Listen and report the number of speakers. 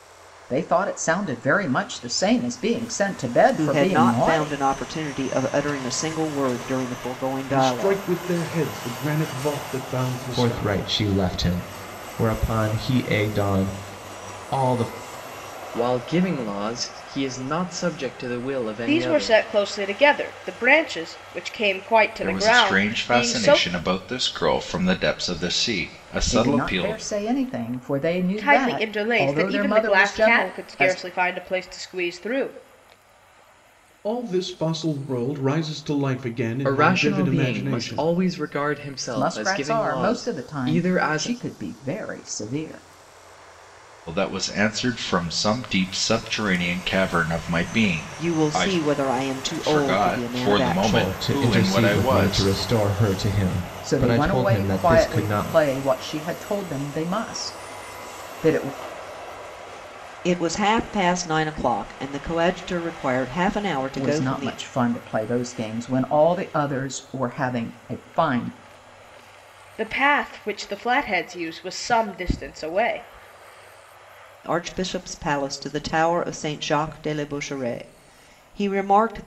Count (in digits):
7